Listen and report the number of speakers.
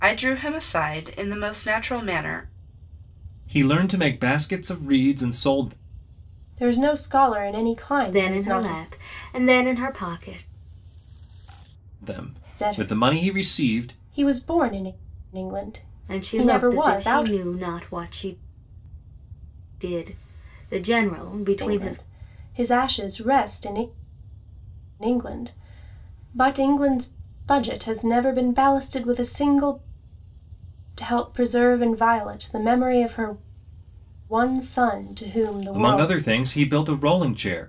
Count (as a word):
four